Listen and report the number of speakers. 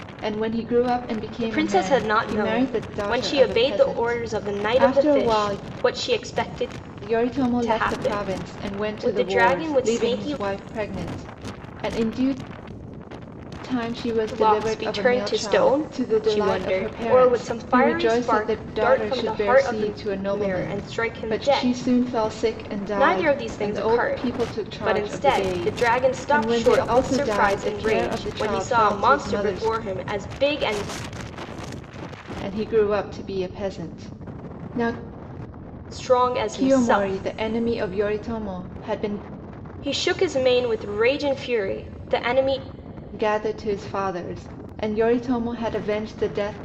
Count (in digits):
2